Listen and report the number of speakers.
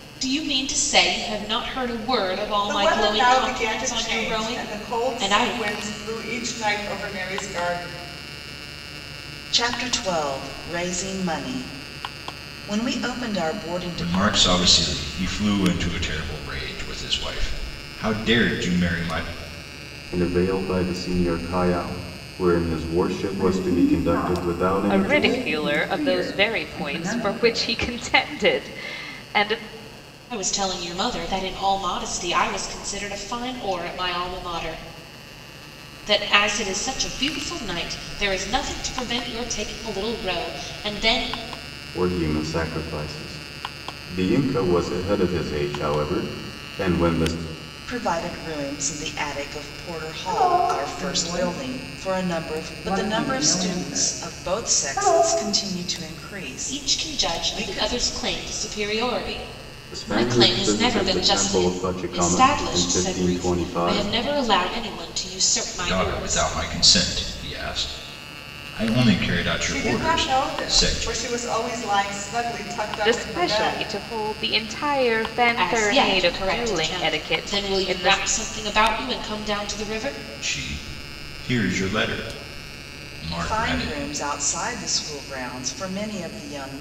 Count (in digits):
7